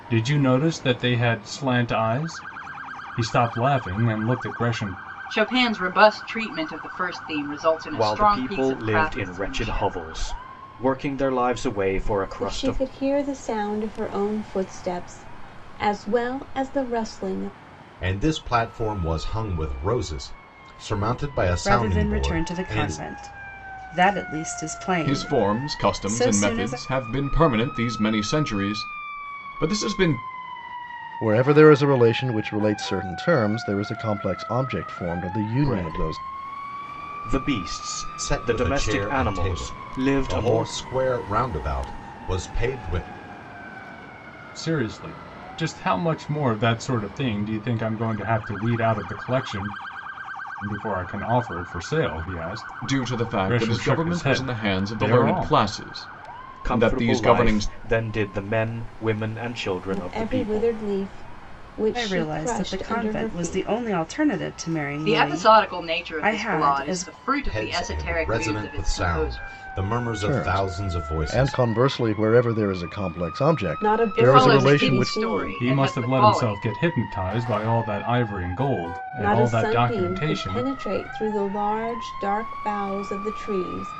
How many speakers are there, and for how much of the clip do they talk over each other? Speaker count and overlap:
eight, about 31%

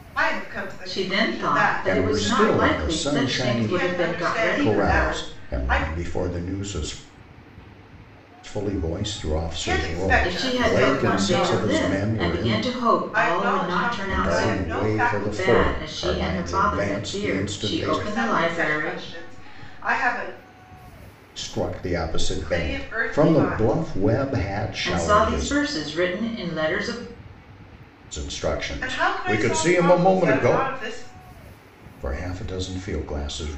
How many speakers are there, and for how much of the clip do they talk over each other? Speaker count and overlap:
three, about 54%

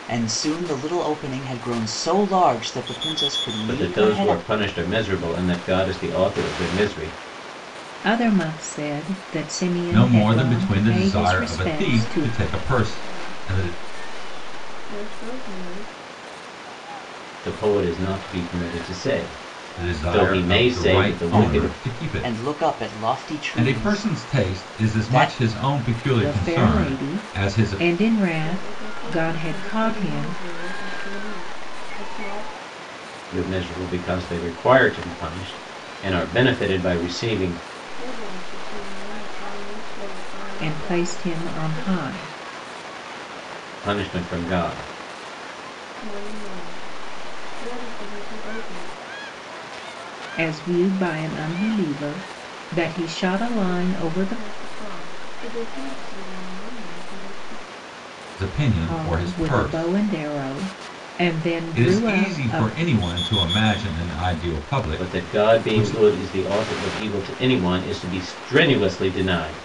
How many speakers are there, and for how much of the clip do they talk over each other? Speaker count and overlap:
five, about 27%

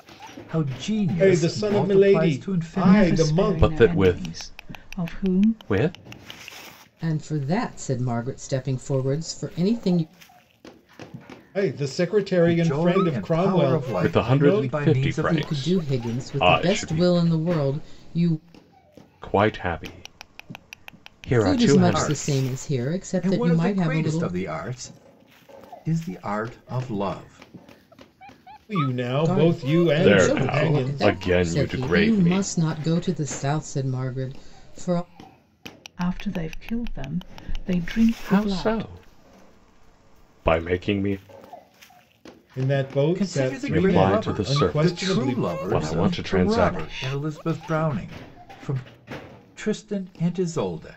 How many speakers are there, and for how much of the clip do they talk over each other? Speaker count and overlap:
five, about 39%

